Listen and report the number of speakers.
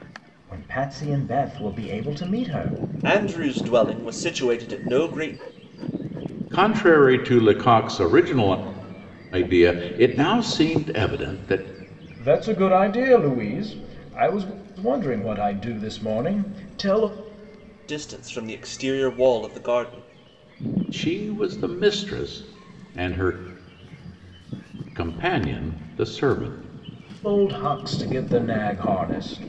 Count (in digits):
3